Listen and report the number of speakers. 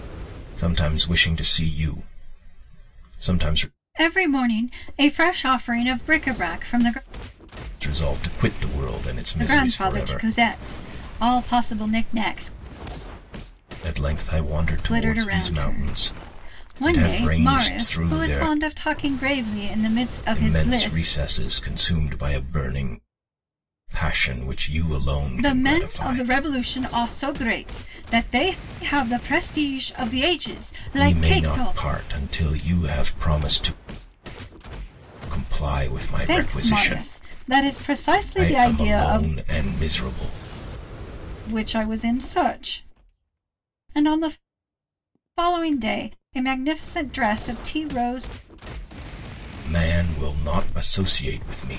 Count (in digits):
2